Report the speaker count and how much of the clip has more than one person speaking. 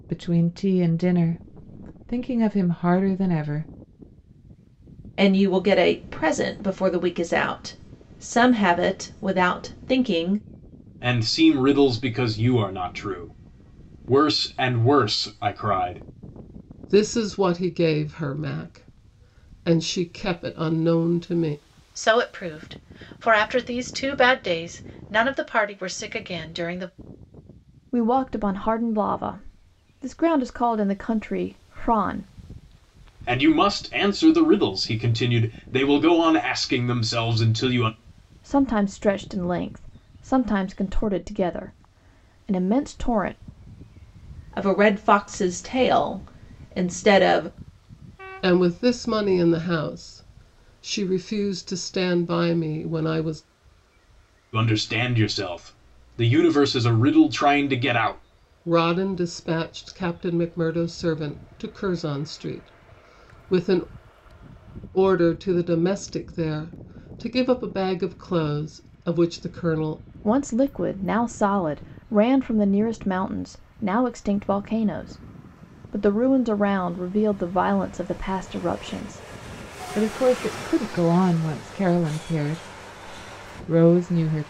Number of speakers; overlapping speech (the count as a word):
six, no overlap